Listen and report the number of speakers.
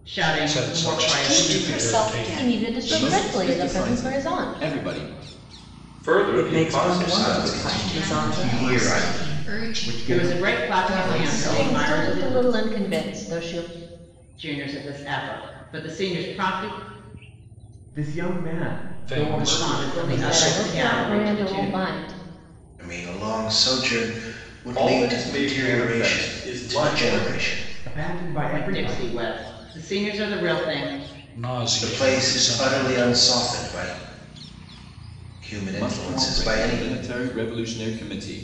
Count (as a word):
ten